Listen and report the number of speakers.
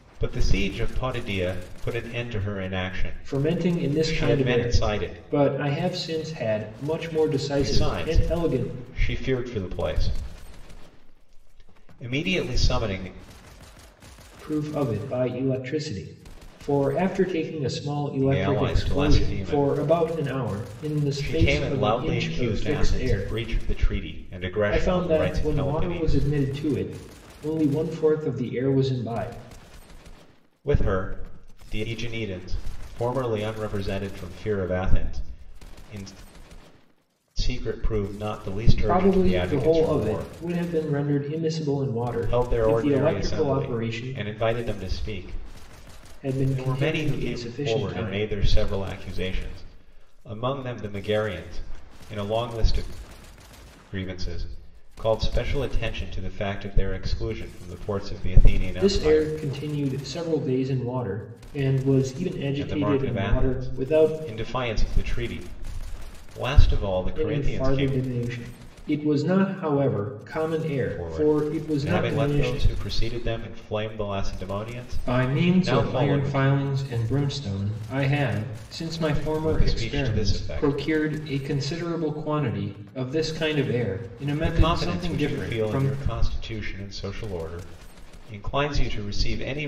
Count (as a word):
two